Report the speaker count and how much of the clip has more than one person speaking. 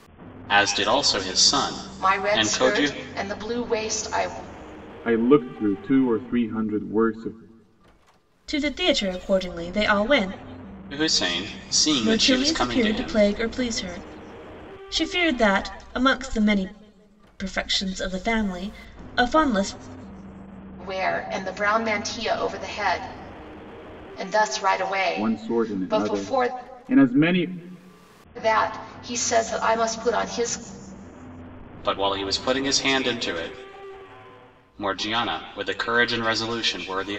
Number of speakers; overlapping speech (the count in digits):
4, about 10%